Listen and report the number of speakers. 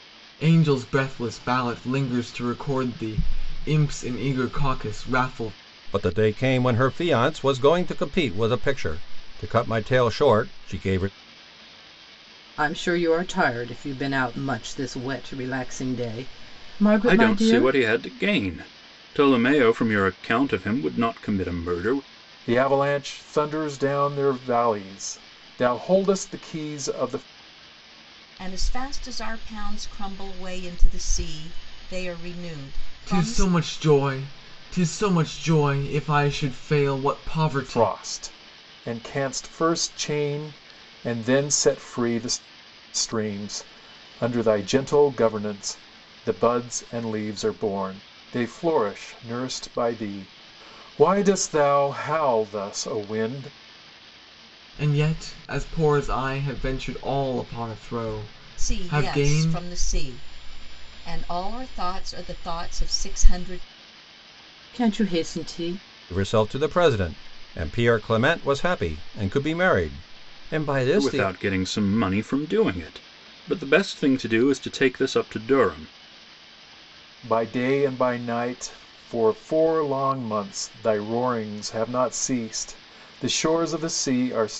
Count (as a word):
six